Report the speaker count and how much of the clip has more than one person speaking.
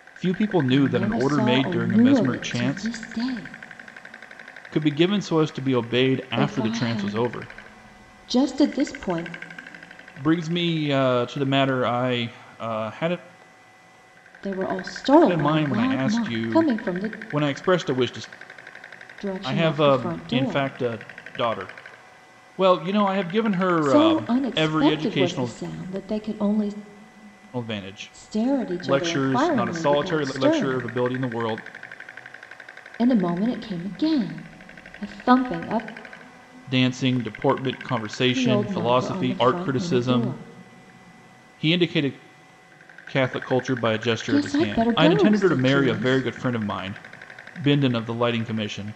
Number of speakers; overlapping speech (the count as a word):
two, about 31%